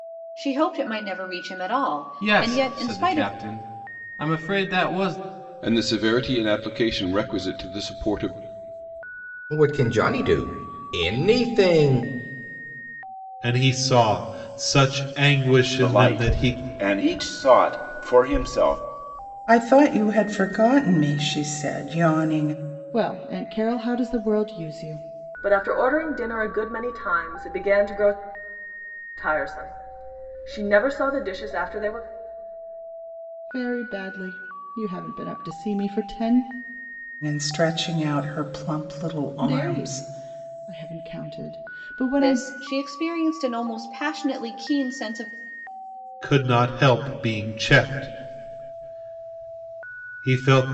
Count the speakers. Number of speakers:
nine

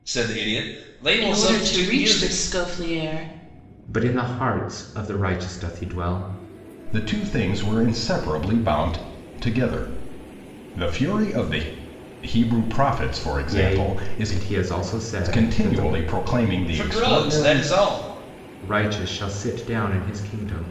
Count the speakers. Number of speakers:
four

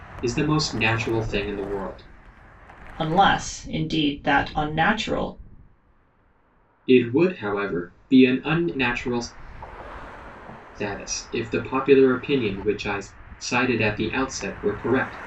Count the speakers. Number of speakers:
two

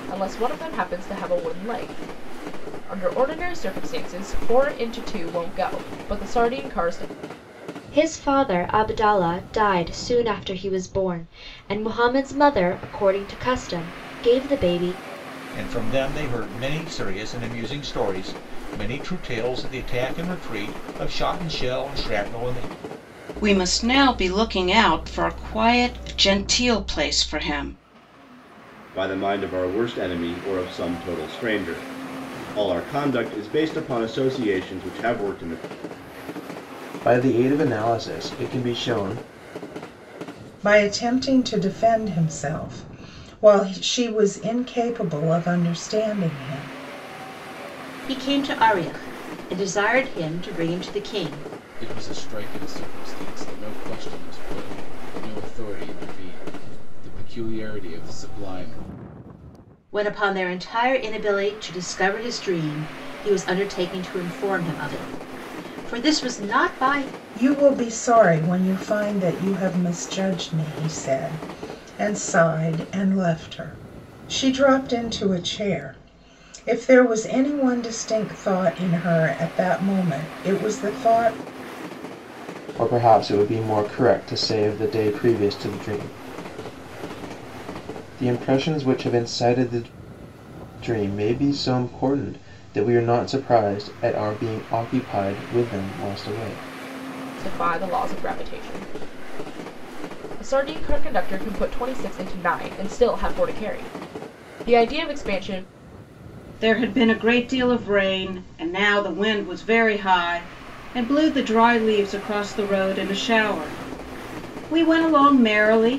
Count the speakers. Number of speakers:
nine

